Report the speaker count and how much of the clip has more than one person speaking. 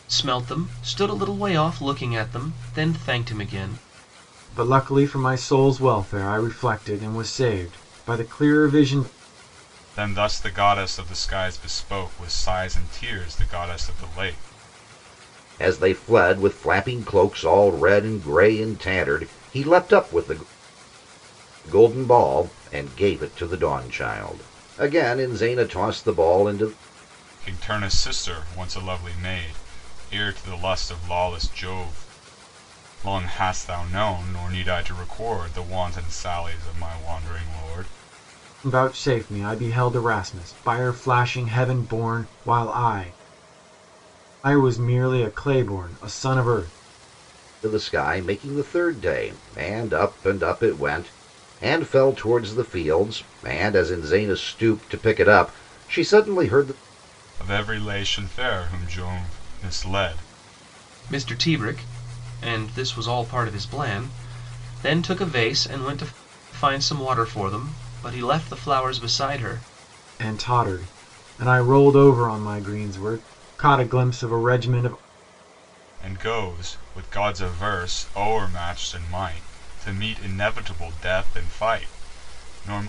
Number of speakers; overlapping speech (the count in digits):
4, no overlap